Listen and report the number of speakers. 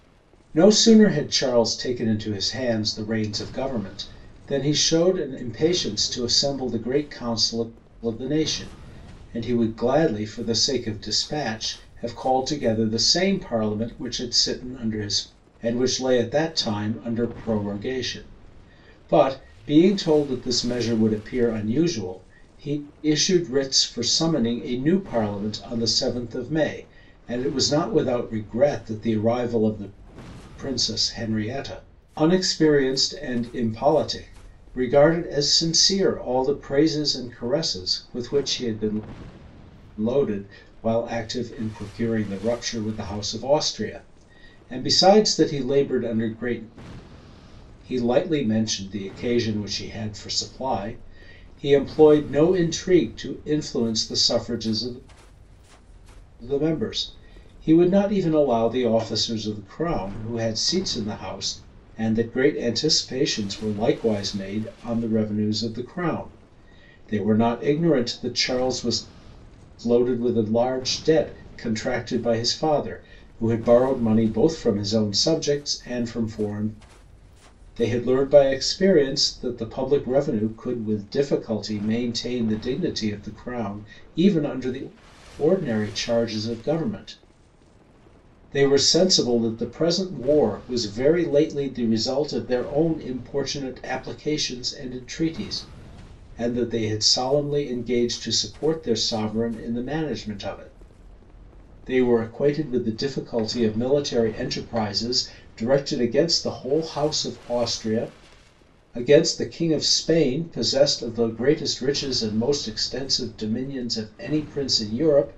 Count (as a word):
one